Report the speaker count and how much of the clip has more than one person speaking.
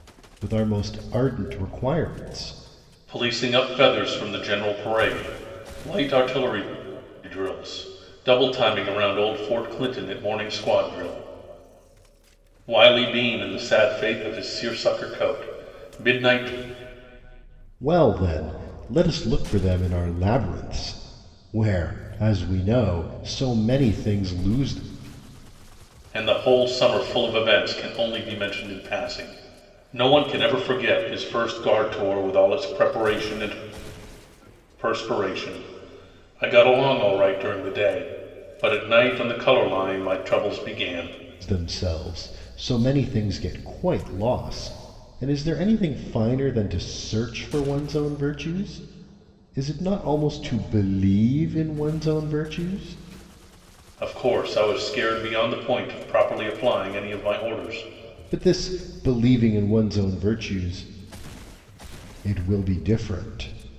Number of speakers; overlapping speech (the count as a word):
two, no overlap